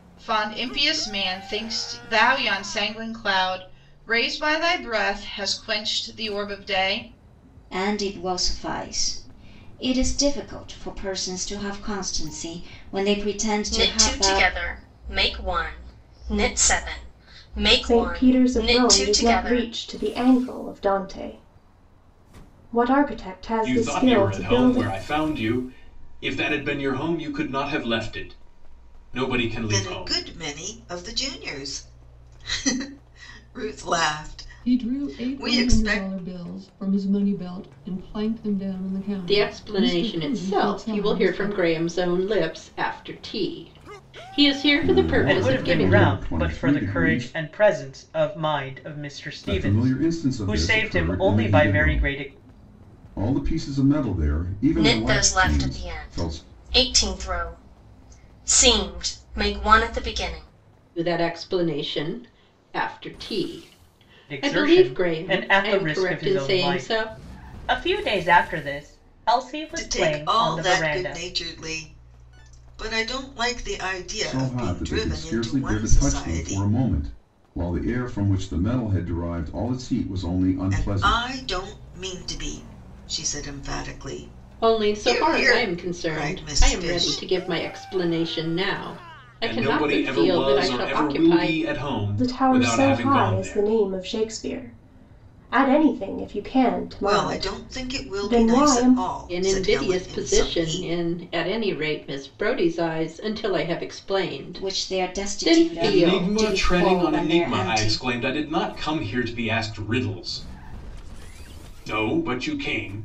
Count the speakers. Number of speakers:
10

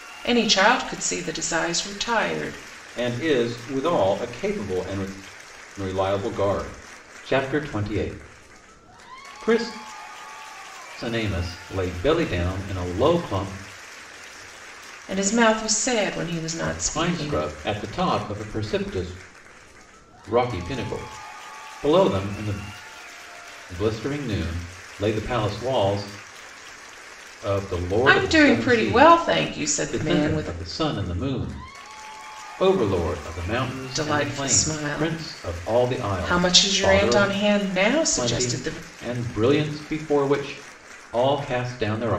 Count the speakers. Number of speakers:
2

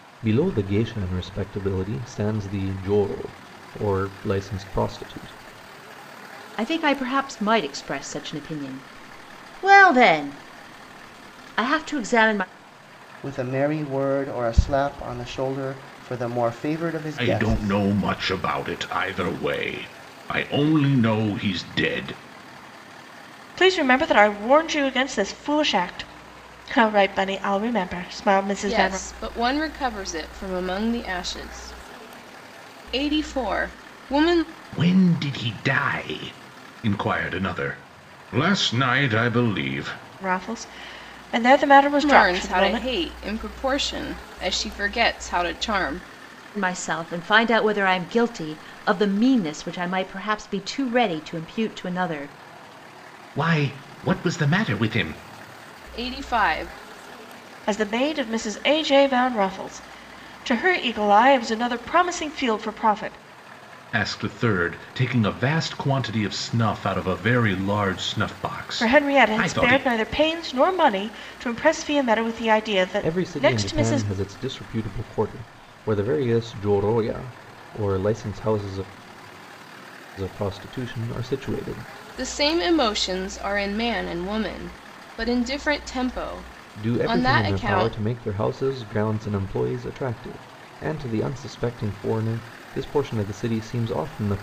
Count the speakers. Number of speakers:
6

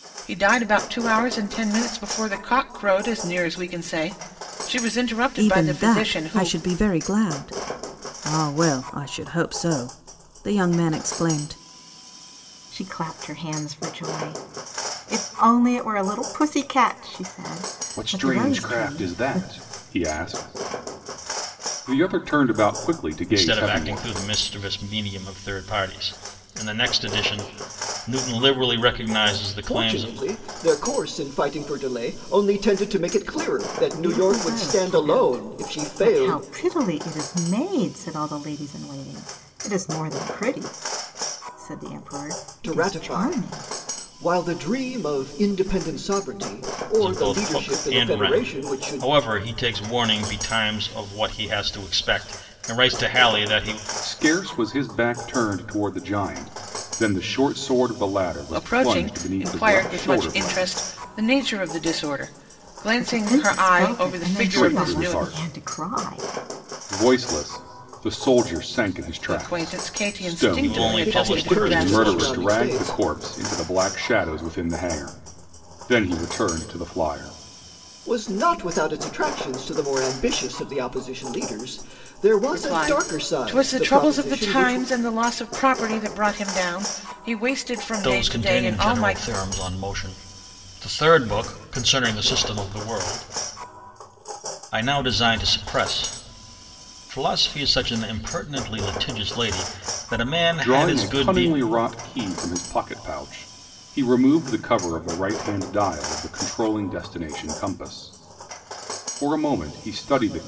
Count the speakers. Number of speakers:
6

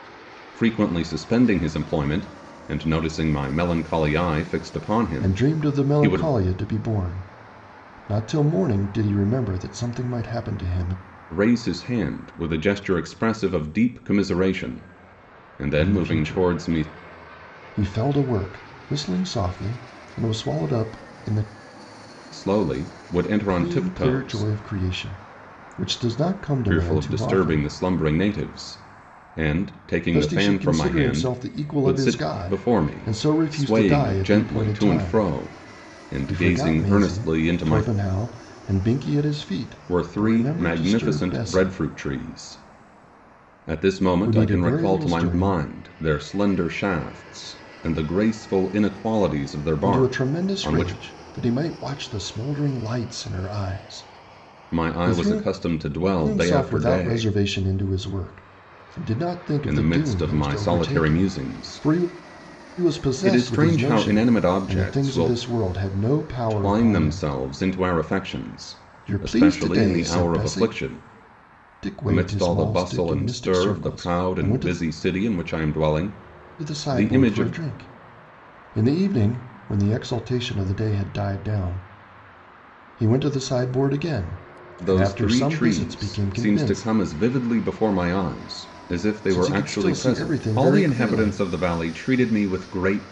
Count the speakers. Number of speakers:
2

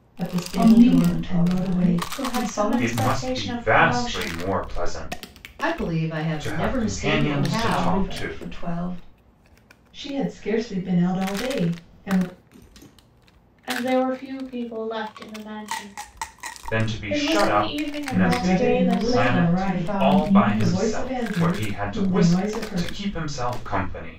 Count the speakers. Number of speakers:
5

